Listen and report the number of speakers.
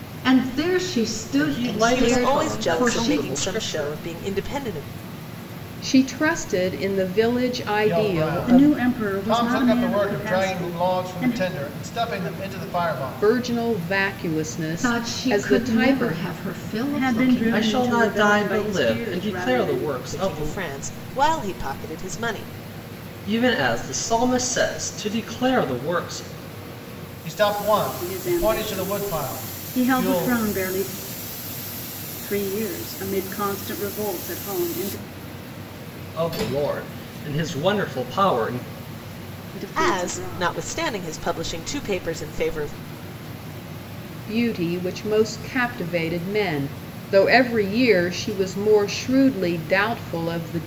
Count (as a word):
six